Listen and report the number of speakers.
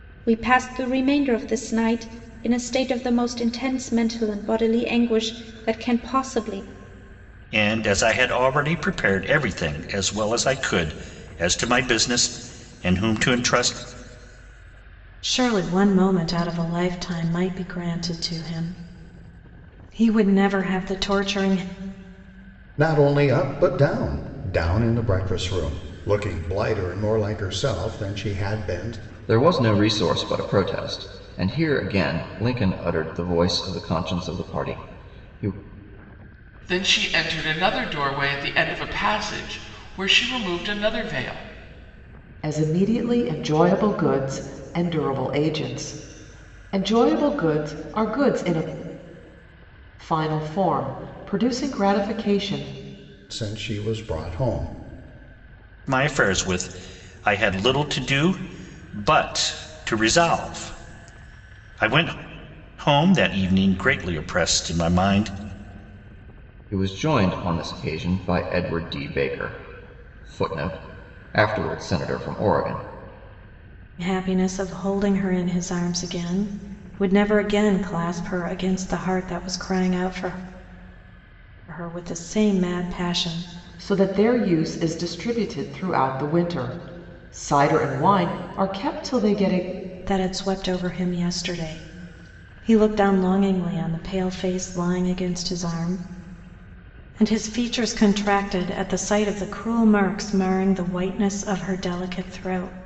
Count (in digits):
7